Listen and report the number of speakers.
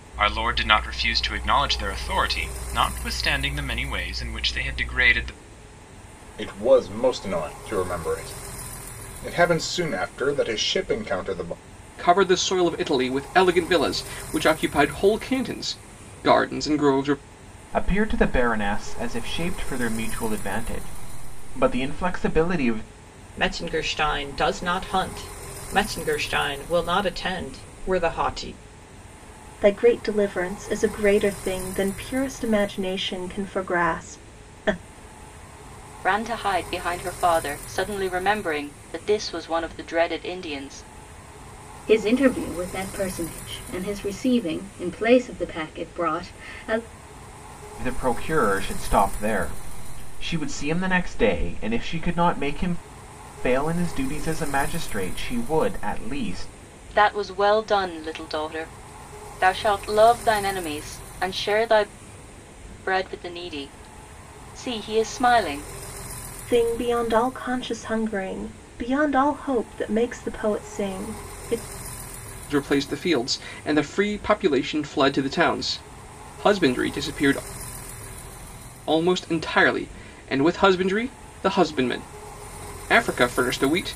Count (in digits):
8